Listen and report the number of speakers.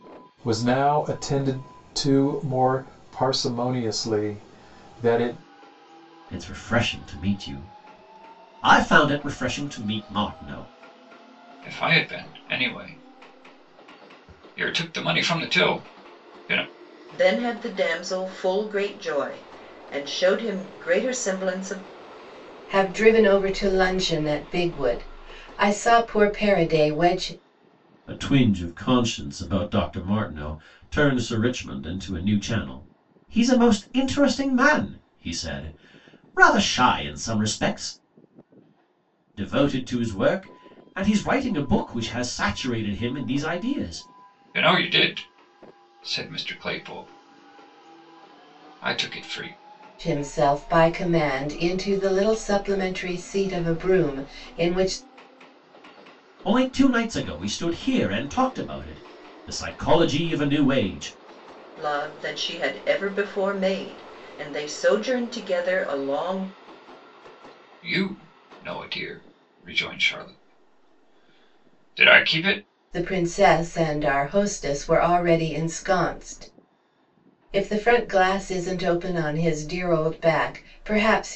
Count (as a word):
five